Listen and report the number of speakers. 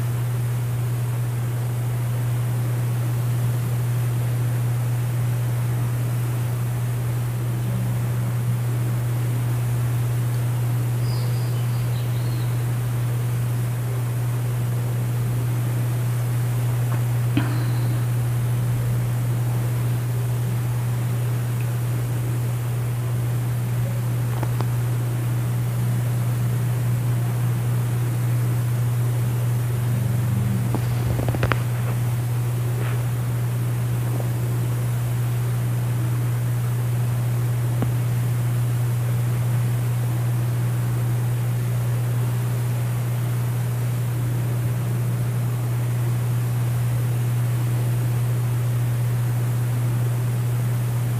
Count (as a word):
zero